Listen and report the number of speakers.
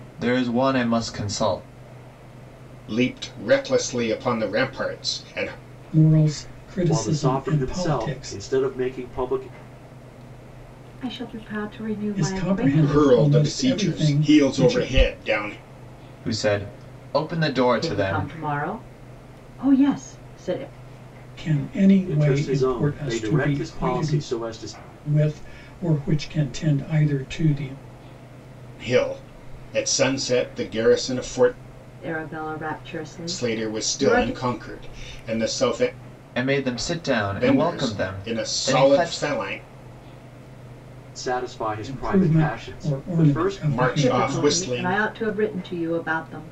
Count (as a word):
five